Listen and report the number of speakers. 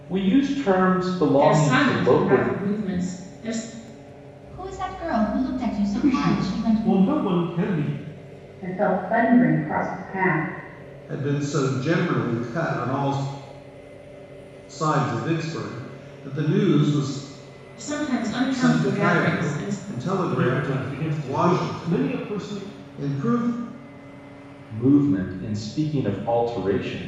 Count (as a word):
six